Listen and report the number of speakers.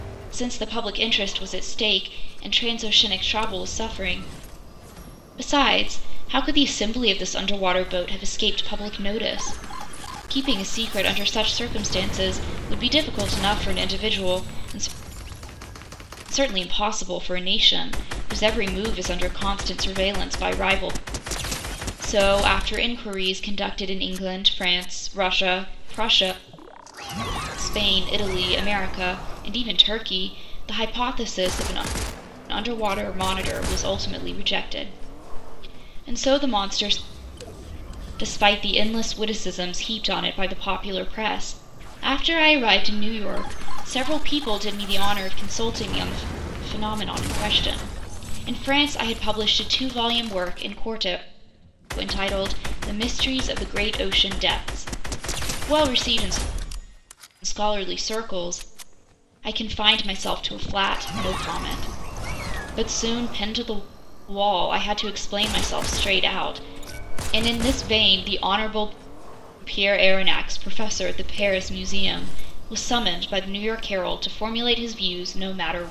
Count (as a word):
one